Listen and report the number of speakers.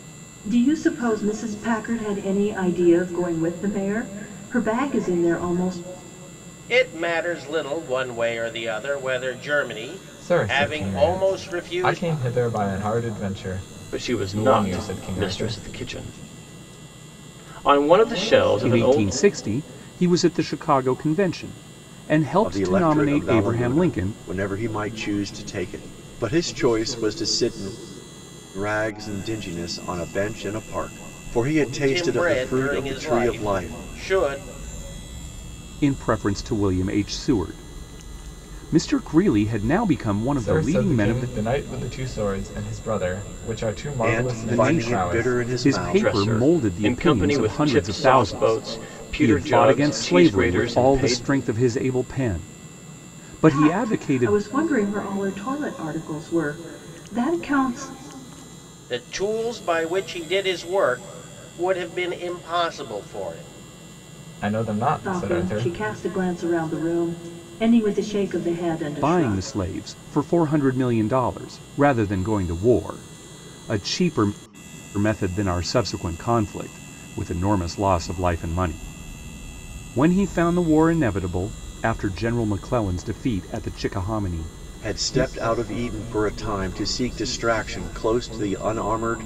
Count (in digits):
6